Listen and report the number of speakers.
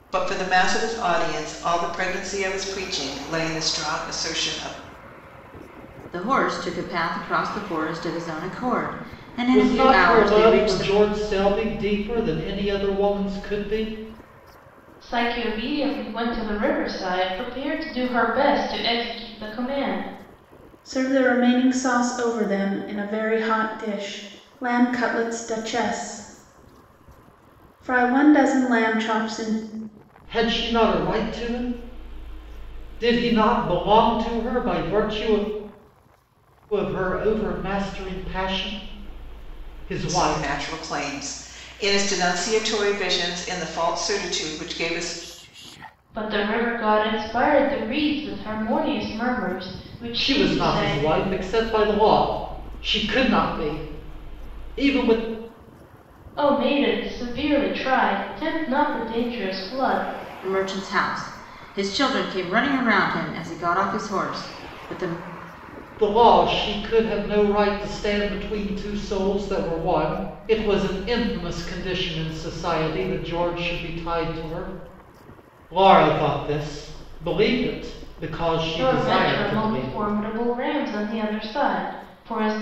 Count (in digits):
5